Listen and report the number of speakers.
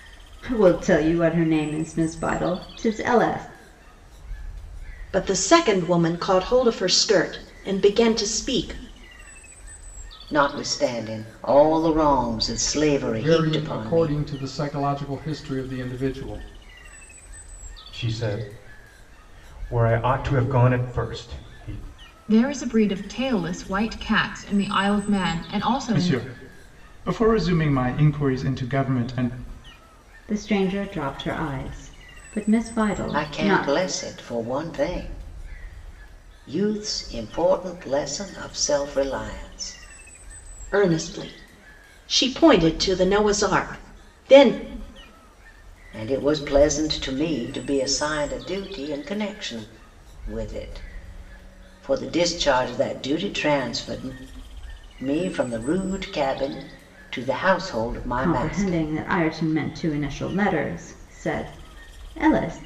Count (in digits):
7